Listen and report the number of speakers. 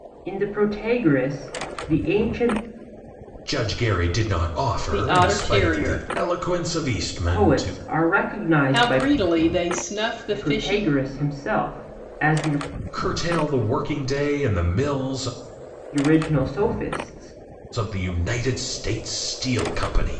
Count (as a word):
three